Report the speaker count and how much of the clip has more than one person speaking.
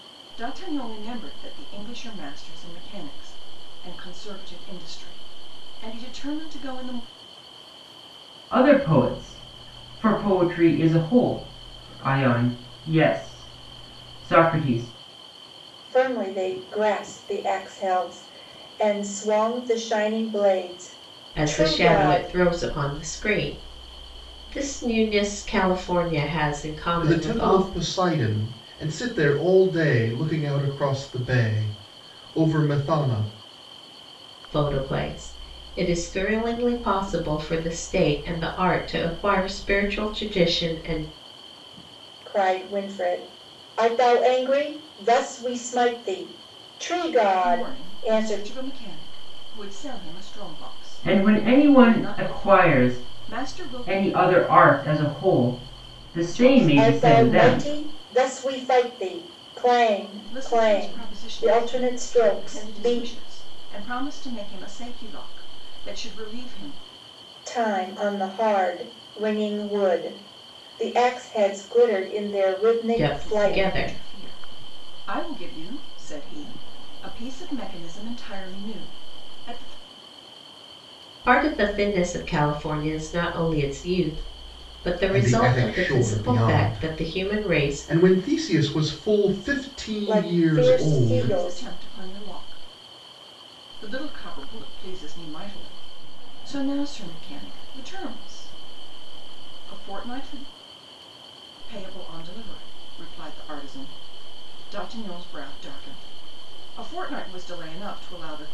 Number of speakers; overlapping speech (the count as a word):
five, about 15%